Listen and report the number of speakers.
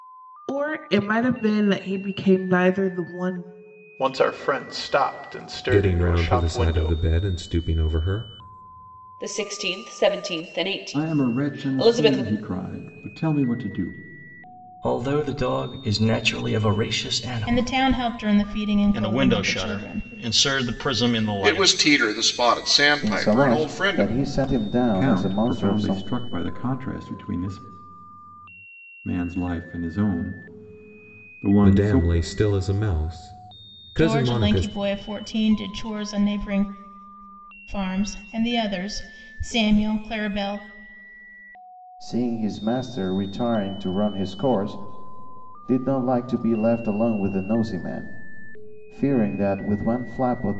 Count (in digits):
10